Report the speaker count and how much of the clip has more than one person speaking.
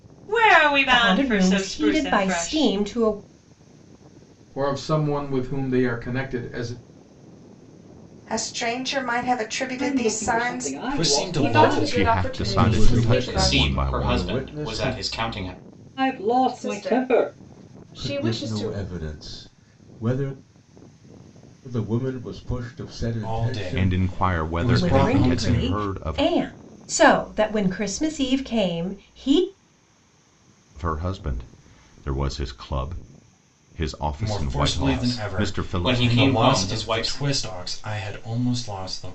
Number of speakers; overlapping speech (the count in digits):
10, about 37%